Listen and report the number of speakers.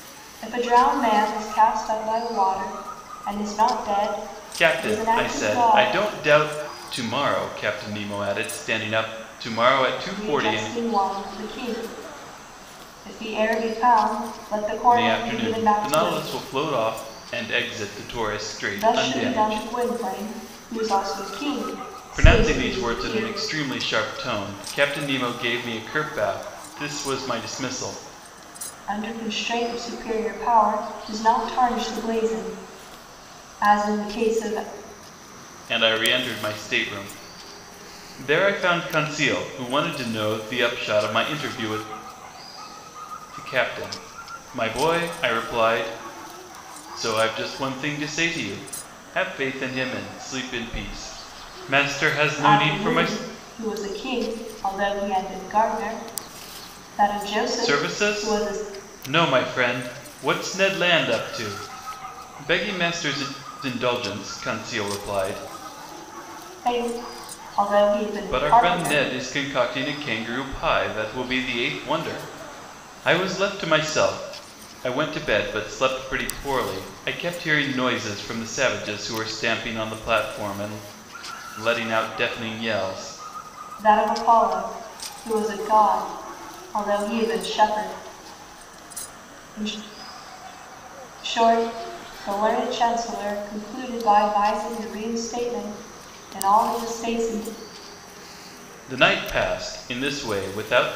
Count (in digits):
2